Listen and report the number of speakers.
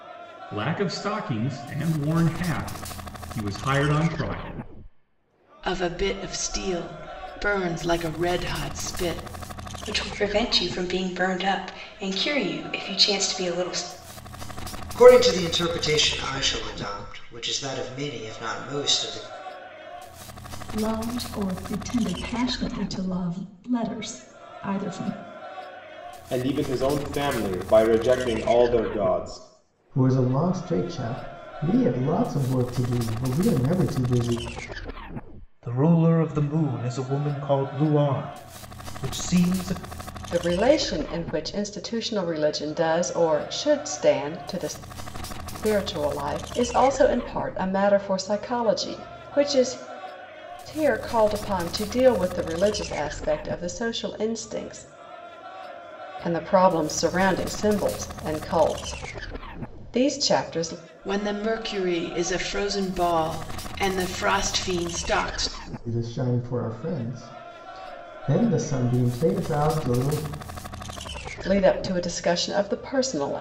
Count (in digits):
9